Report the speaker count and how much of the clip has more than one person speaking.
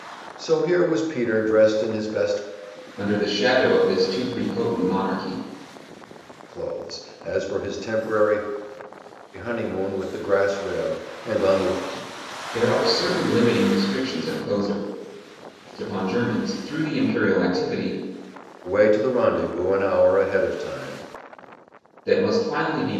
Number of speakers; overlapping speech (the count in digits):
2, no overlap